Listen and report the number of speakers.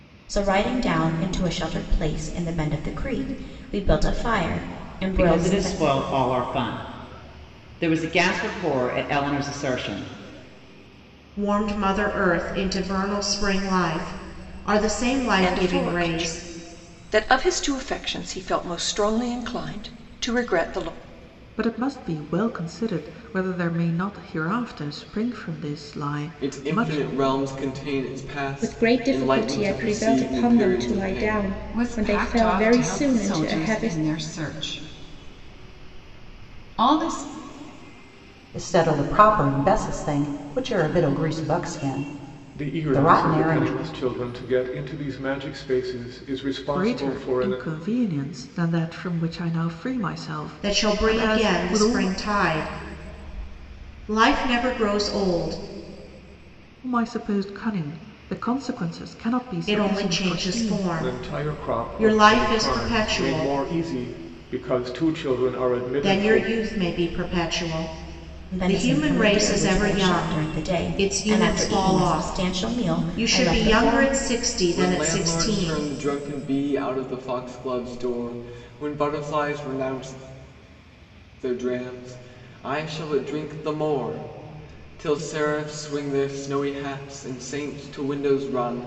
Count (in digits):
10